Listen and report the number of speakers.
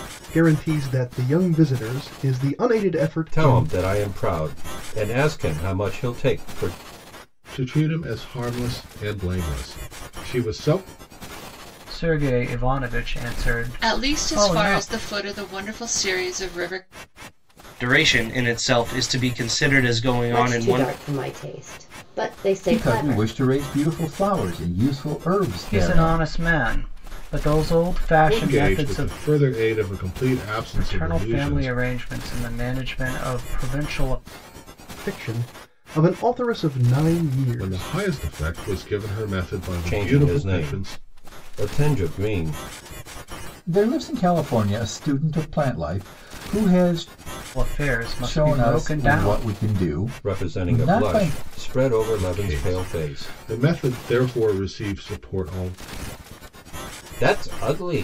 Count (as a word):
eight